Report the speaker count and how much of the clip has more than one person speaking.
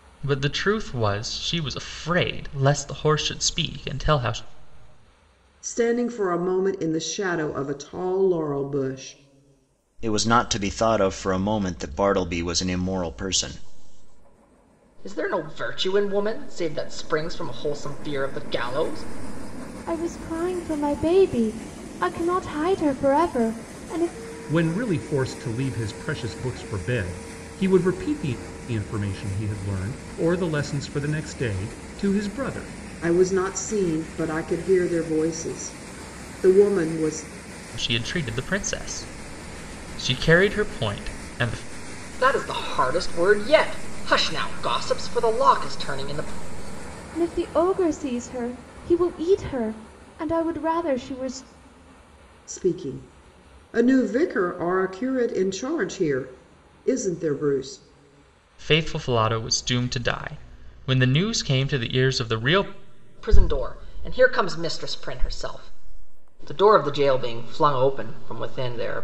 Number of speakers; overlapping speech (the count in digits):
6, no overlap